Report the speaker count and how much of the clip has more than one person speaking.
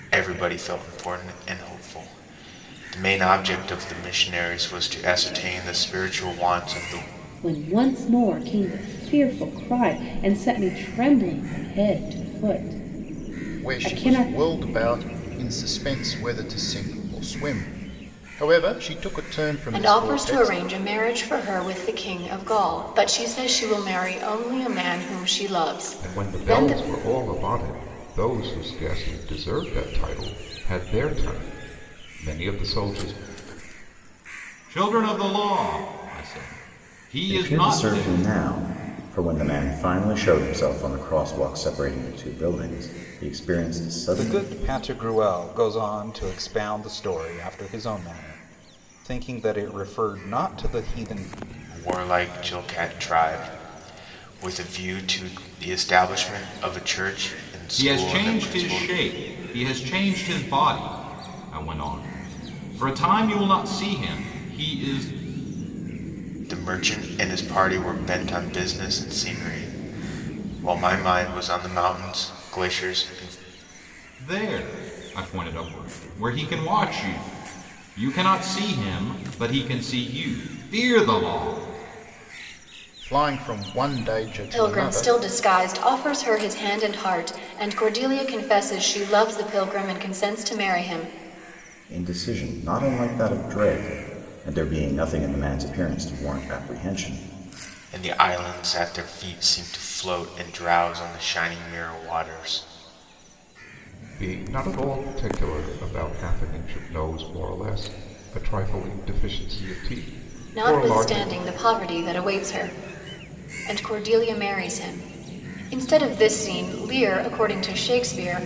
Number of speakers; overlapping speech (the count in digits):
8, about 6%